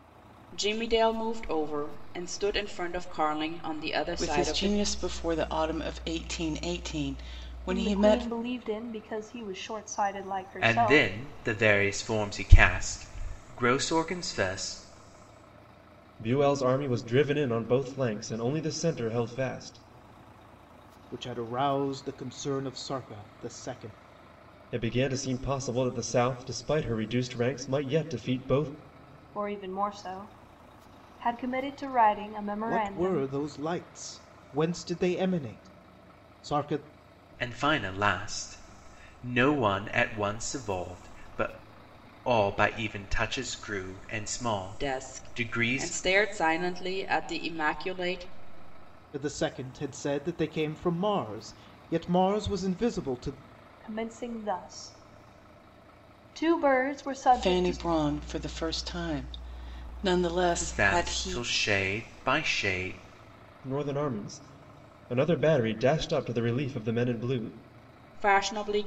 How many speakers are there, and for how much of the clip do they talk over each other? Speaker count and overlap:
six, about 7%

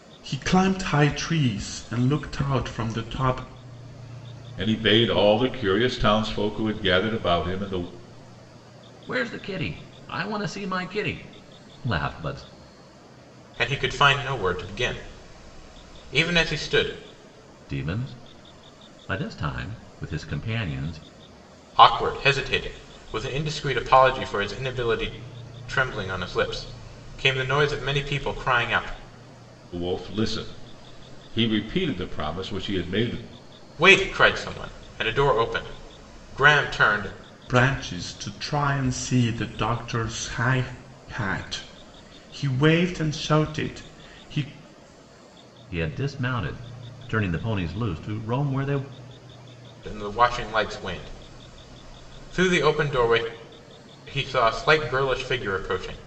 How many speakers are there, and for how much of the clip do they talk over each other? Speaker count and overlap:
four, no overlap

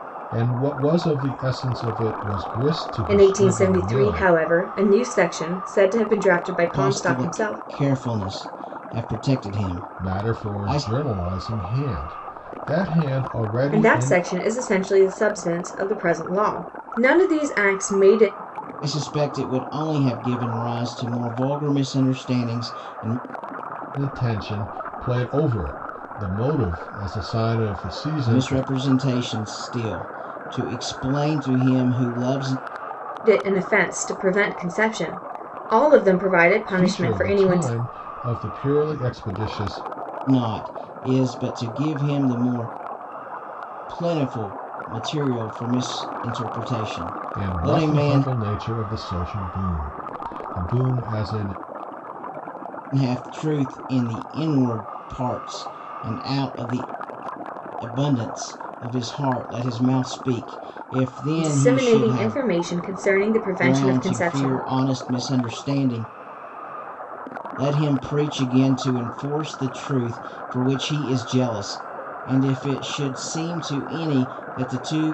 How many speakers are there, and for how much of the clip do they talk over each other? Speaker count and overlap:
three, about 11%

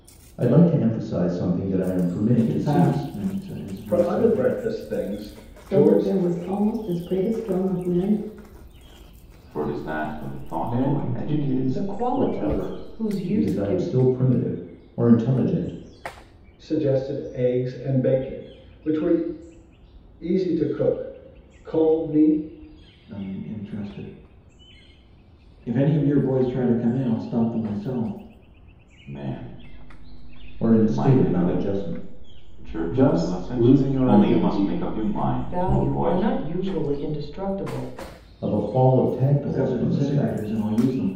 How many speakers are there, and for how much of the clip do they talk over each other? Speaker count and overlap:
seven, about 23%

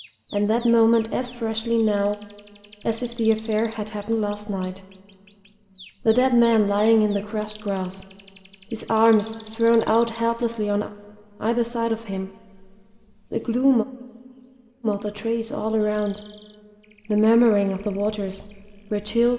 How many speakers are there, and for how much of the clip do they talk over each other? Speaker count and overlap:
one, no overlap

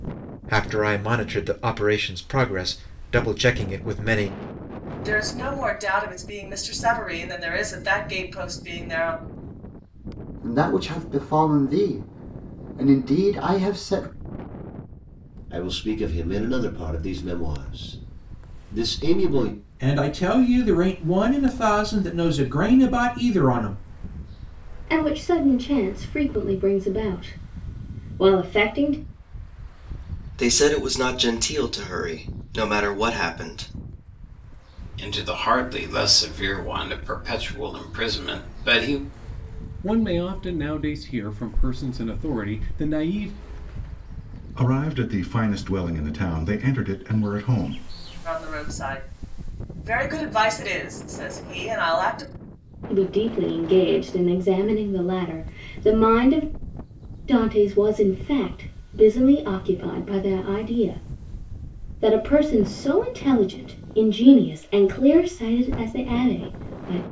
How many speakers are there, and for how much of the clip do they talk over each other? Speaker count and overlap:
ten, no overlap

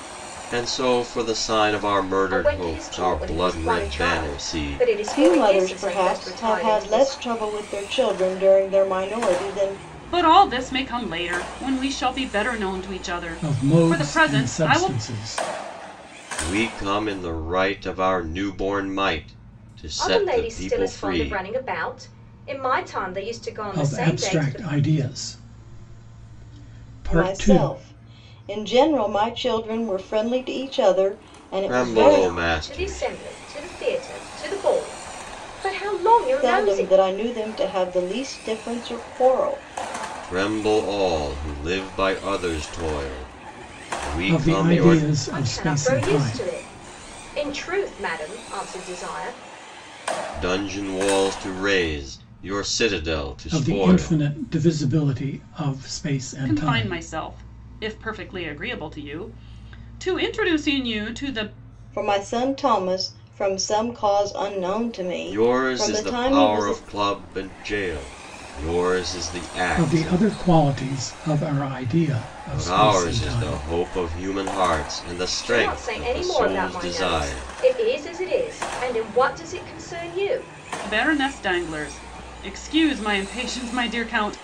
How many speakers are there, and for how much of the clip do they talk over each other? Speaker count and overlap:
five, about 24%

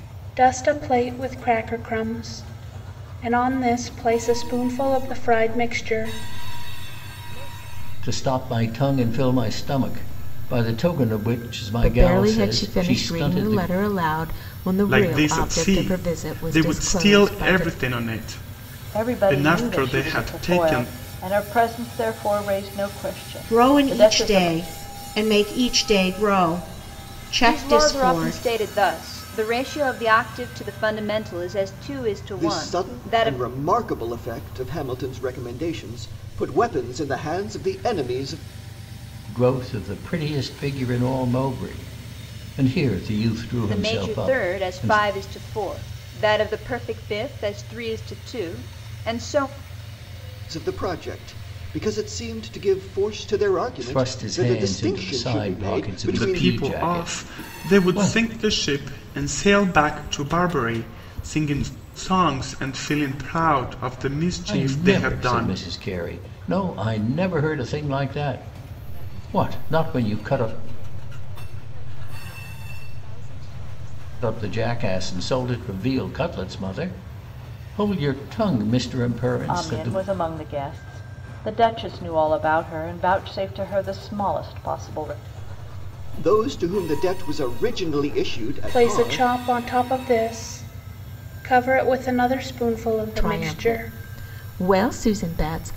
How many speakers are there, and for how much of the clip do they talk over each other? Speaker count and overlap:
nine, about 29%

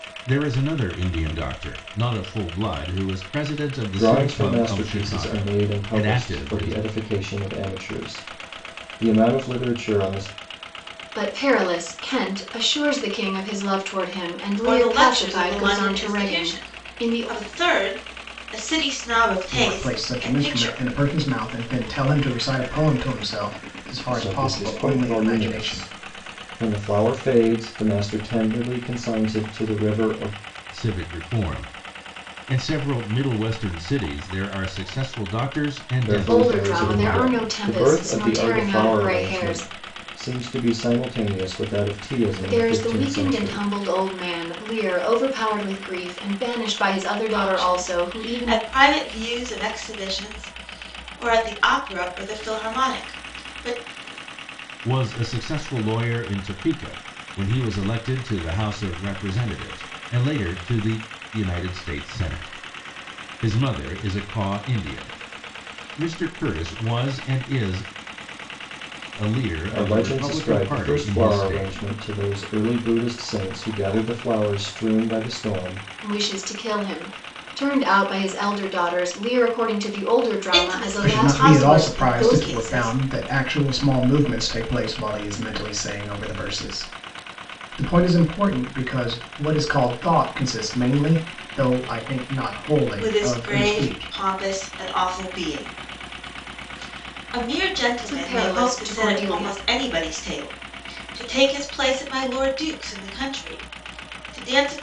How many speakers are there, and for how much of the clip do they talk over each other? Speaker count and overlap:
five, about 21%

